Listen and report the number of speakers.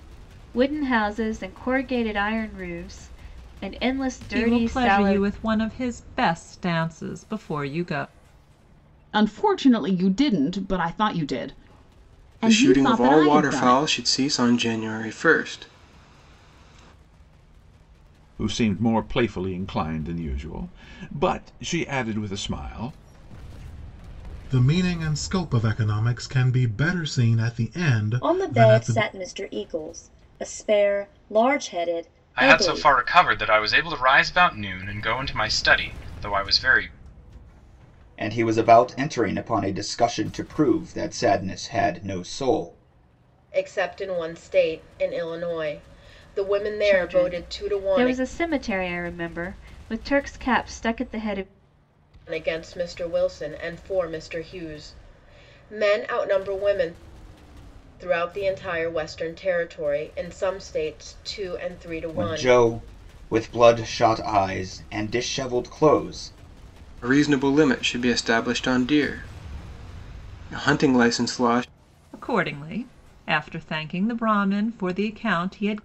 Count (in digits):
10